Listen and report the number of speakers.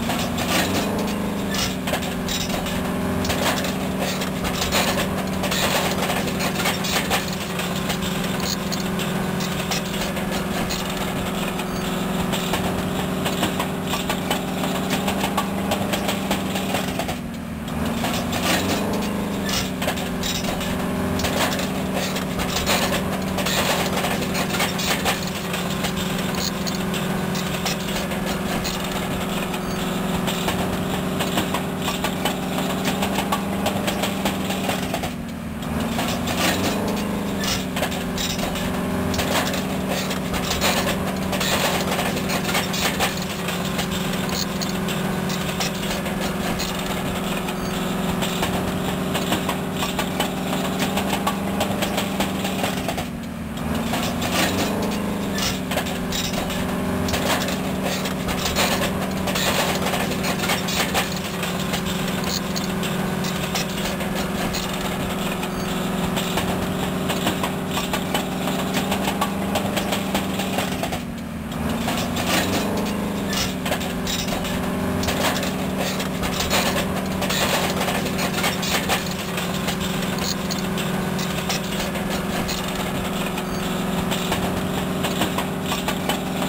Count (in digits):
0